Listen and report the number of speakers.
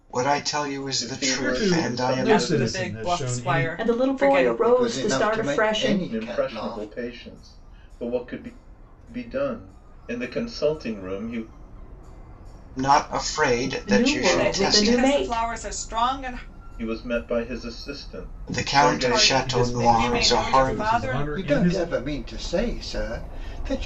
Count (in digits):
6